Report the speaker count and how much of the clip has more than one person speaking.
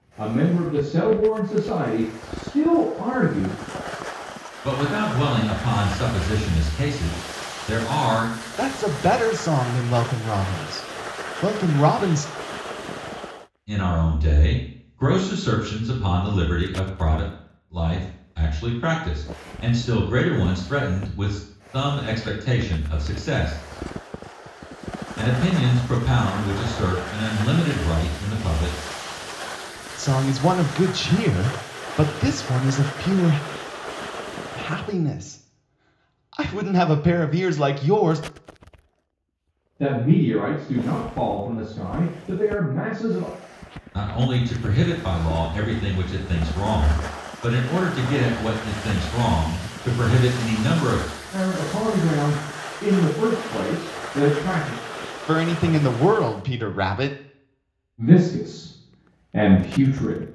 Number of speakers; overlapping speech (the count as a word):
three, no overlap